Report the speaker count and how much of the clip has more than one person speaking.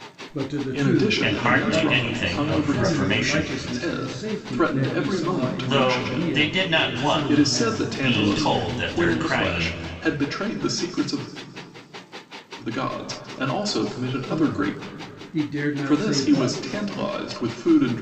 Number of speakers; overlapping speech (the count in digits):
3, about 58%